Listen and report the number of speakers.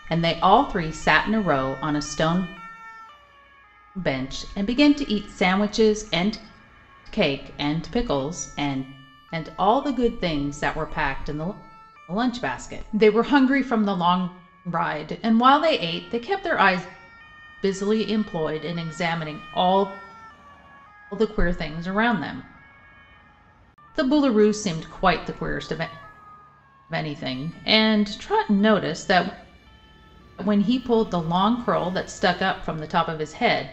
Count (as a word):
one